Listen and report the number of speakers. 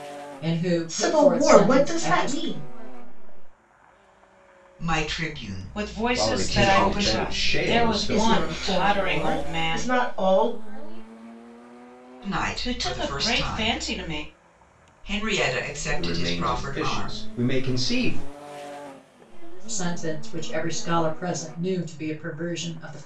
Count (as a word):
six